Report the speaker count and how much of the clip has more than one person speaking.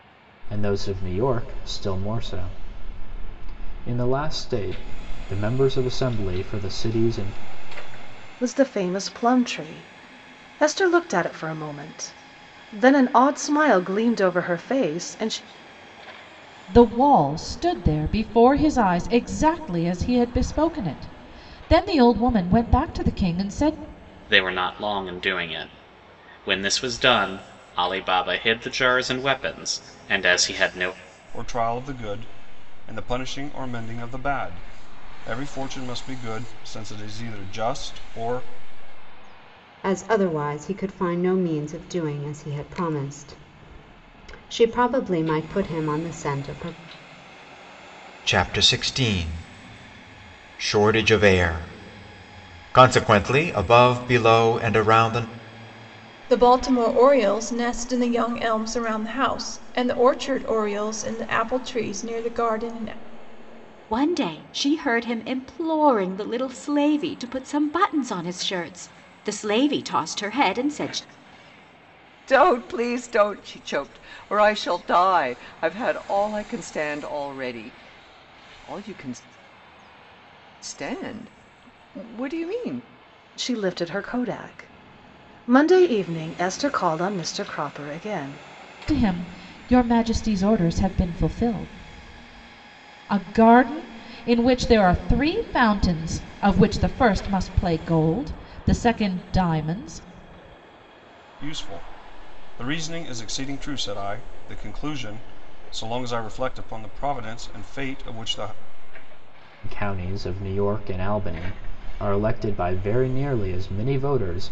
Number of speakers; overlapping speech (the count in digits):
10, no overlap